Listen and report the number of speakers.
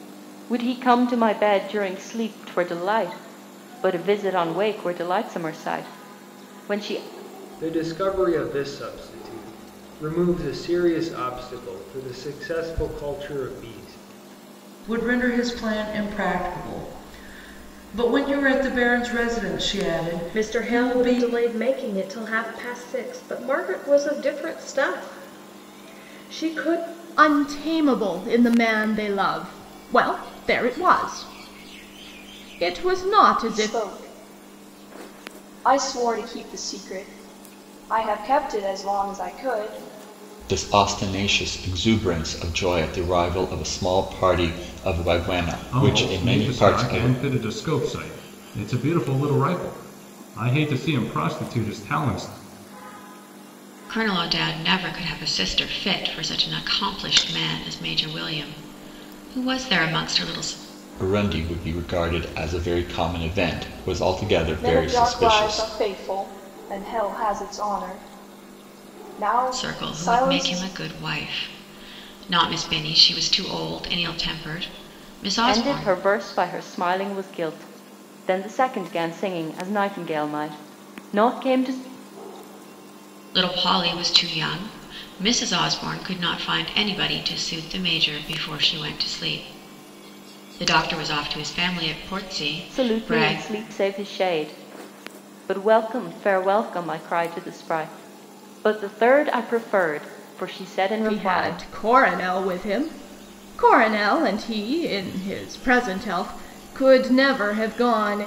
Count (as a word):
nine